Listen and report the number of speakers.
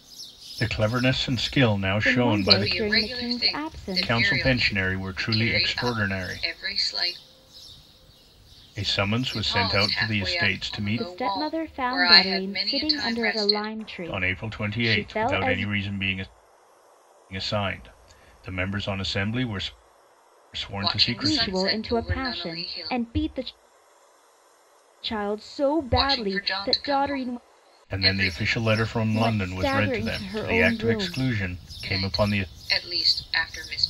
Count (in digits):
3